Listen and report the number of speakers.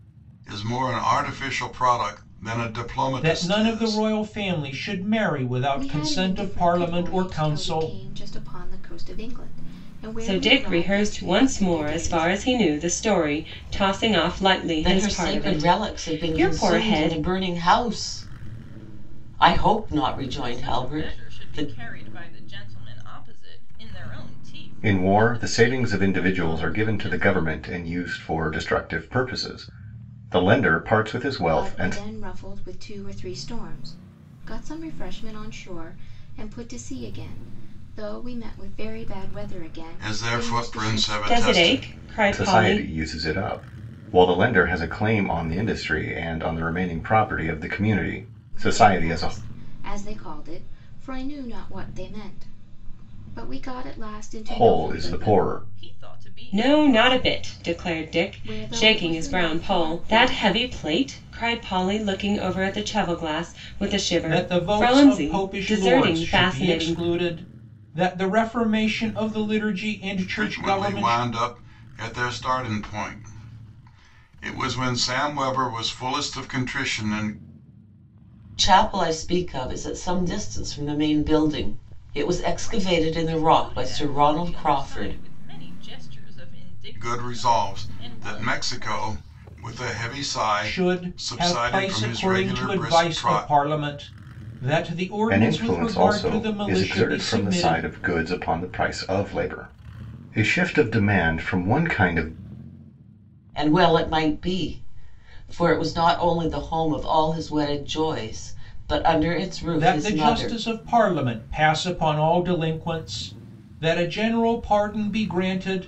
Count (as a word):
seven